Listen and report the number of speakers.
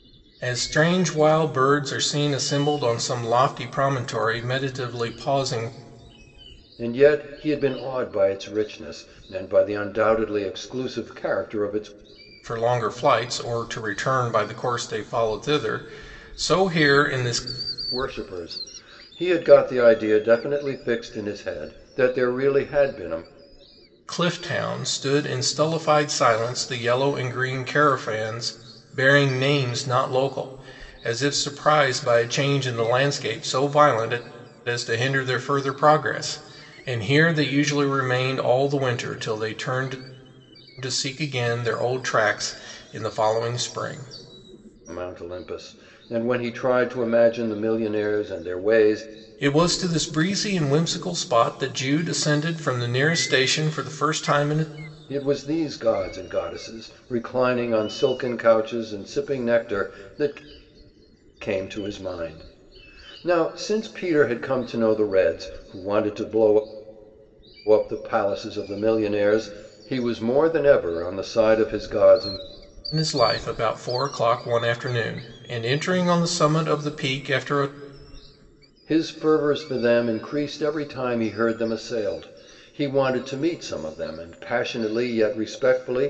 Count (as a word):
two